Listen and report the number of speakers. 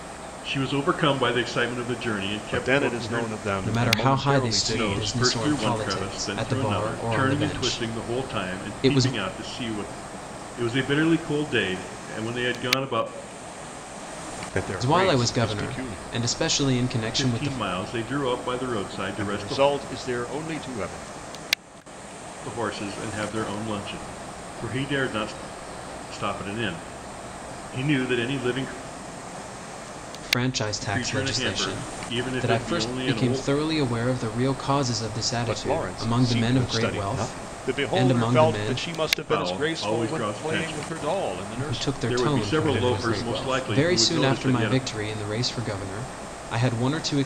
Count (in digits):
3